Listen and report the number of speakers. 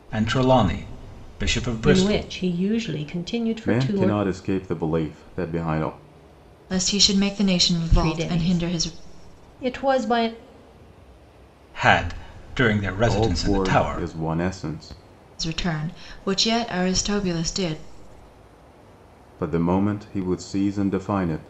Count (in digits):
4